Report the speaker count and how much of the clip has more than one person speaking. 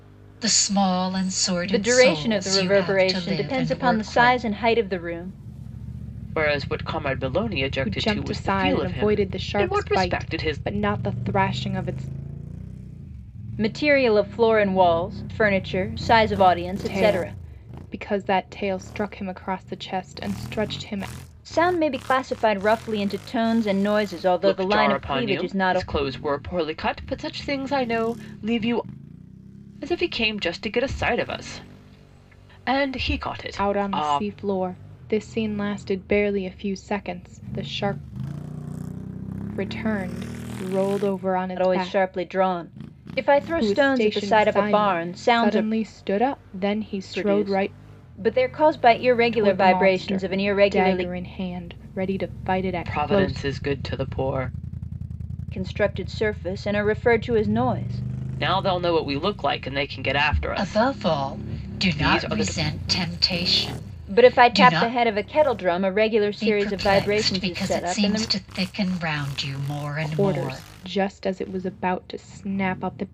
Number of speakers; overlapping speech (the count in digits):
4, about 28%